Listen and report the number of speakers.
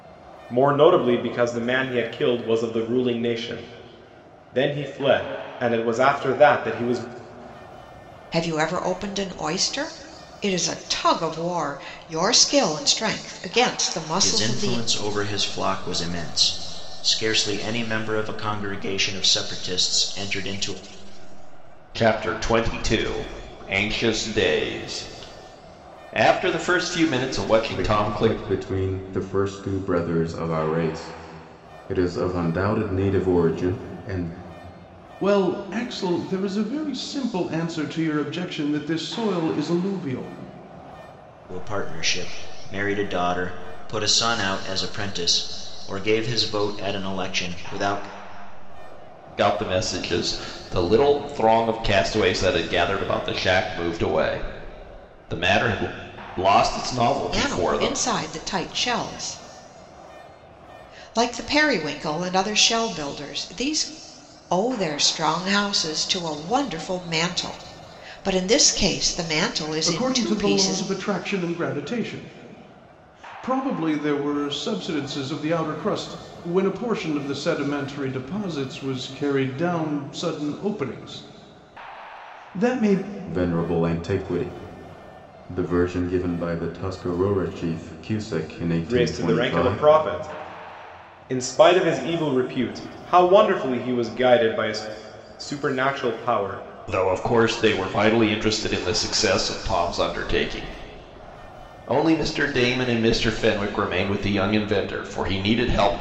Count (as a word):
six